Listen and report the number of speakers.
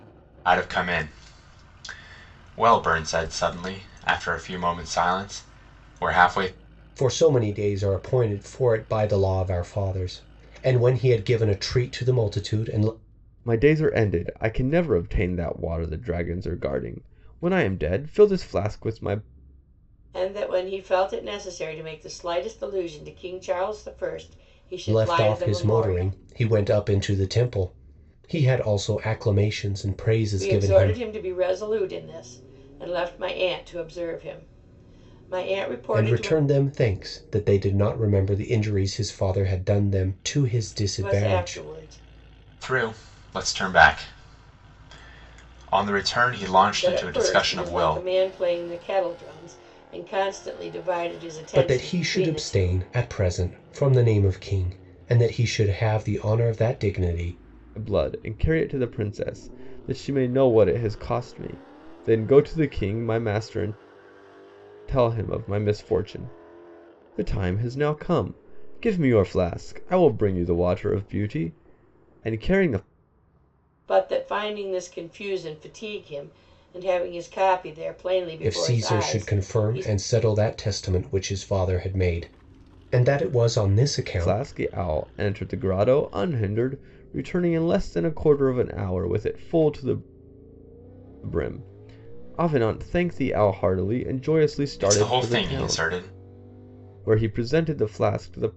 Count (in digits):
4